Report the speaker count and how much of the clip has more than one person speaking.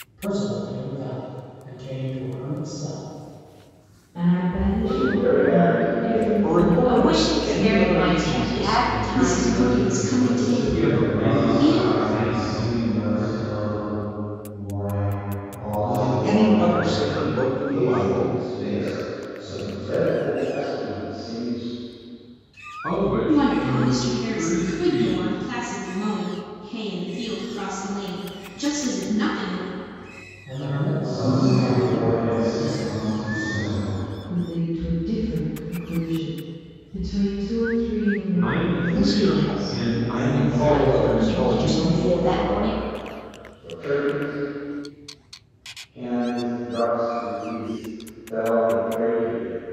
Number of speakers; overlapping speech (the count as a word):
nine, about 42%